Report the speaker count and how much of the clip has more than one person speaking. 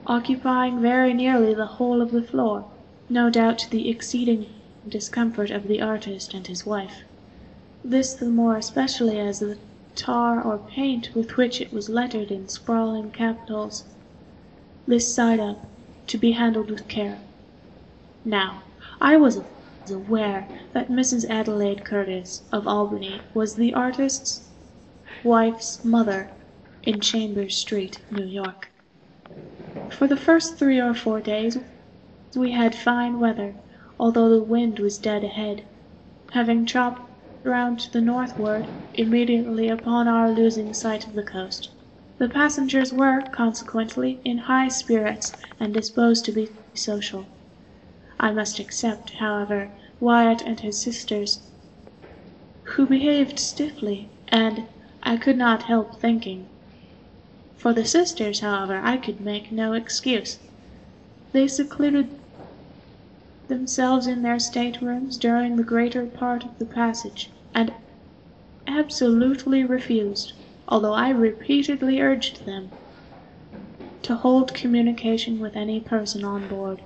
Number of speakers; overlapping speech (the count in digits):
1, no overlap